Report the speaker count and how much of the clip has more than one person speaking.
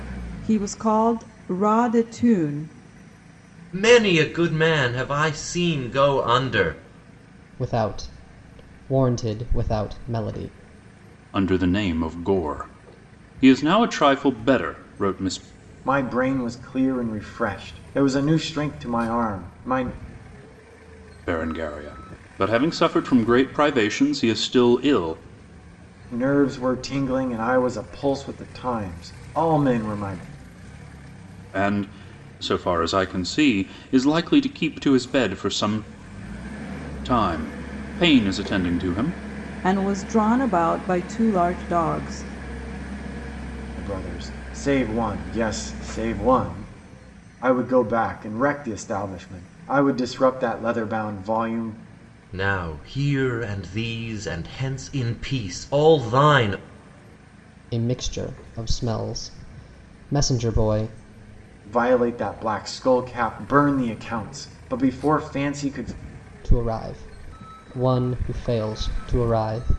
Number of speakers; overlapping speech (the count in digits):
5, no overlap